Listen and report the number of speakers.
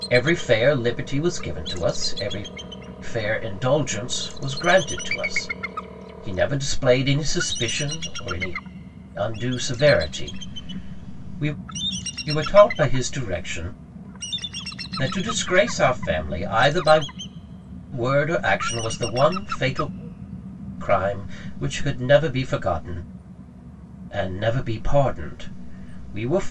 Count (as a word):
one